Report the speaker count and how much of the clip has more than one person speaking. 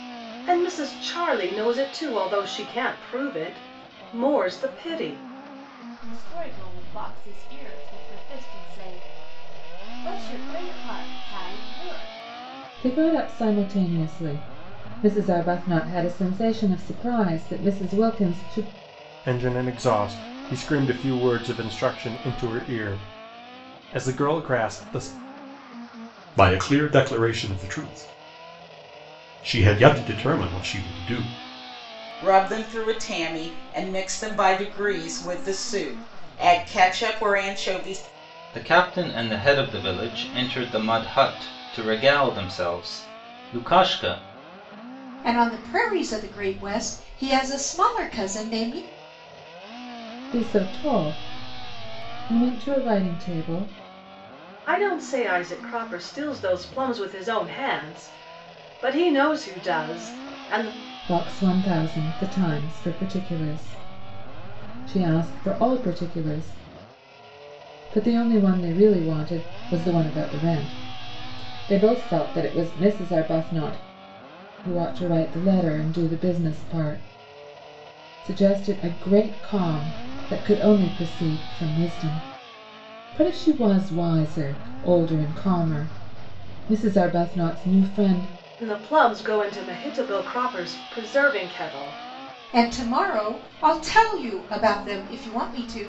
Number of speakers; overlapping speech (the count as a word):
eight, no overlap